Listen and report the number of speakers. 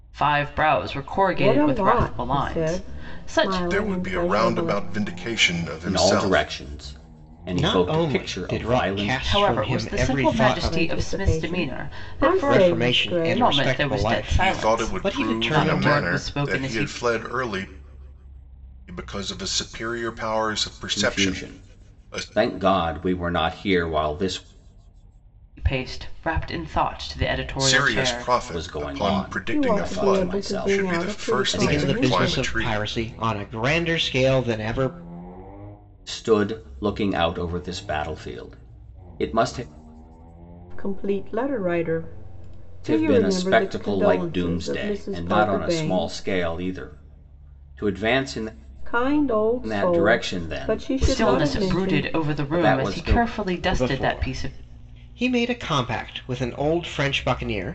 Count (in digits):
5